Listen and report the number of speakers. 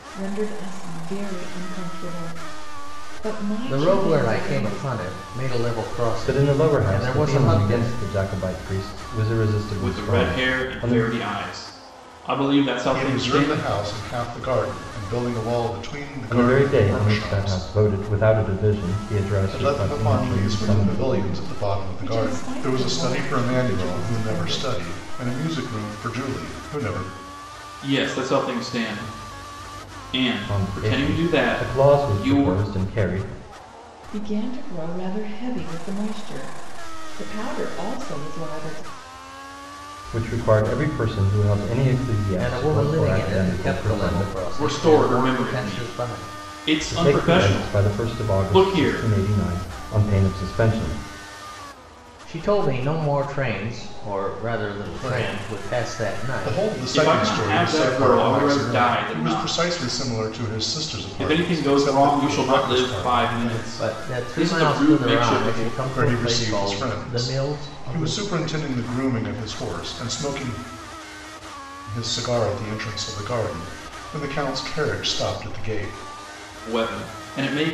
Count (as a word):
five